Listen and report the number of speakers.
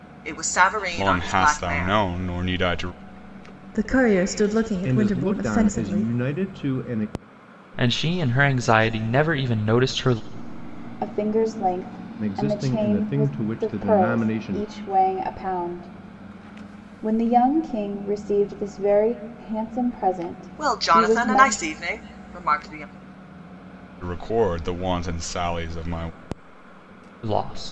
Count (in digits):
6